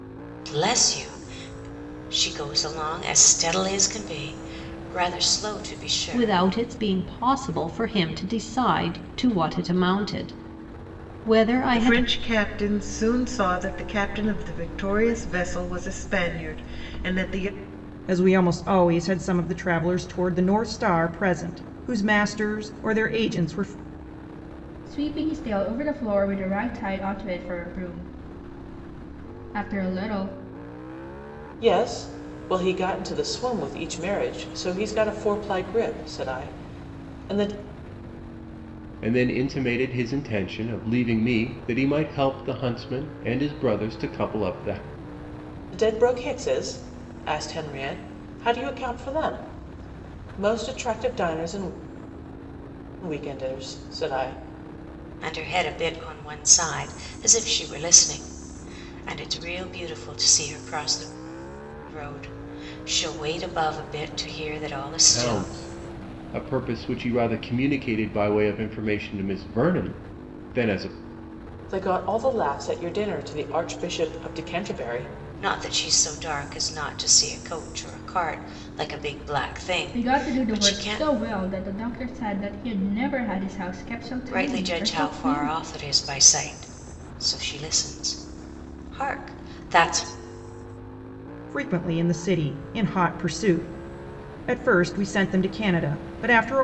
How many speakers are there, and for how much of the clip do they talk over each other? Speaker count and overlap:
7, about 4%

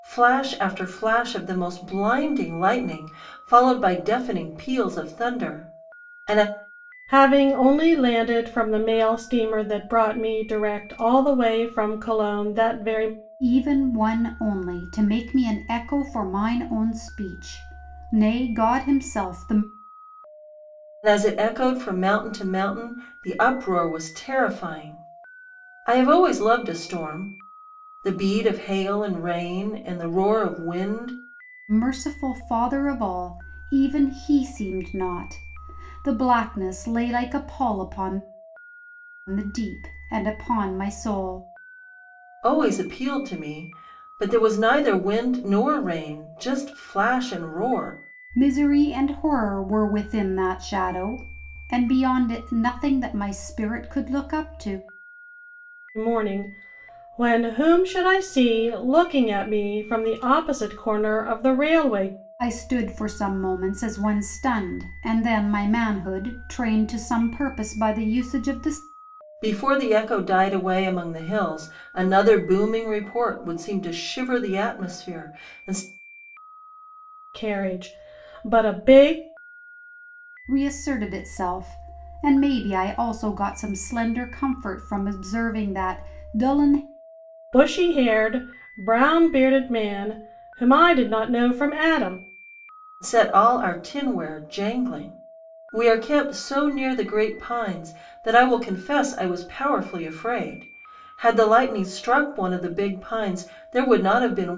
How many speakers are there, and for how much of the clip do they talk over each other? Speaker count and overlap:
3, no overlap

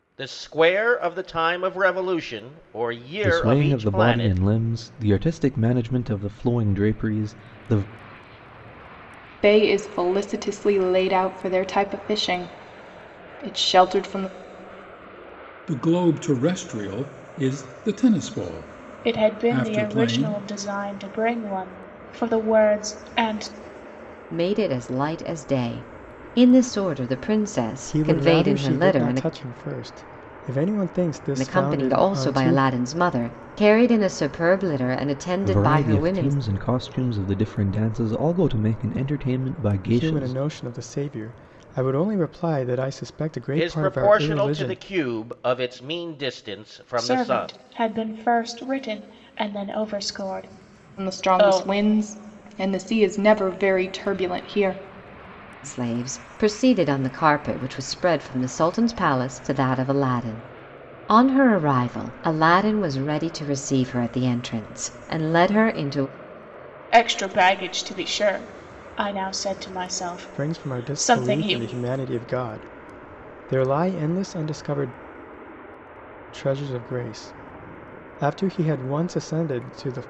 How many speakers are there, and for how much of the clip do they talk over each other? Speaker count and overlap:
7, about 13%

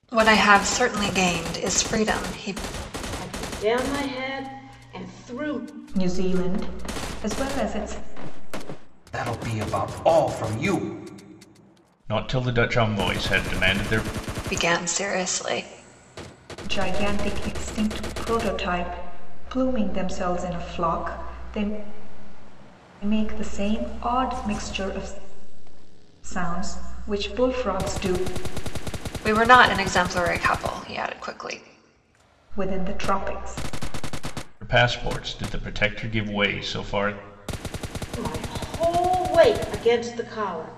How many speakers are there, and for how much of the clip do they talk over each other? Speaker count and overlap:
5, no overlap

